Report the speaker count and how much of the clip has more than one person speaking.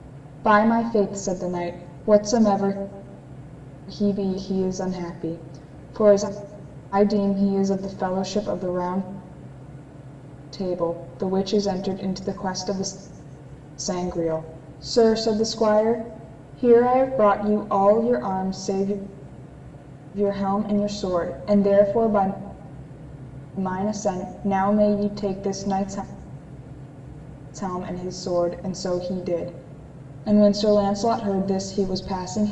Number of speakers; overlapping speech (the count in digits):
1, no overlap